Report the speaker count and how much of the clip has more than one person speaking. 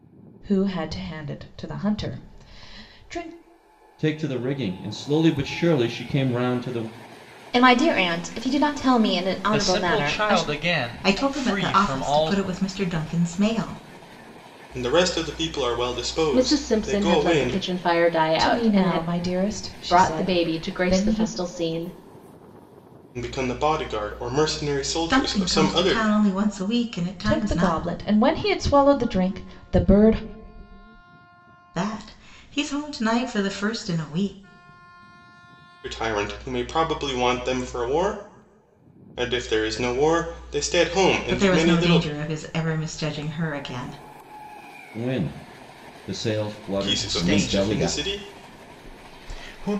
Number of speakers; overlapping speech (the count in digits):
7, about 20%